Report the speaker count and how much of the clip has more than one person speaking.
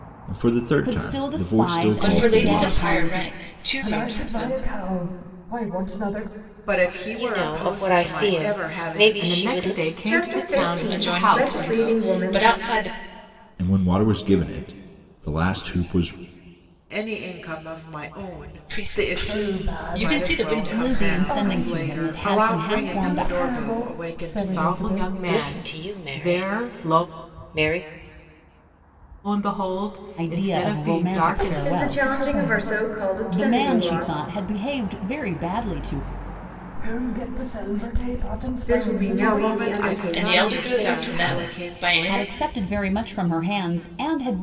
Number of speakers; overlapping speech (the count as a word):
eight, about 54%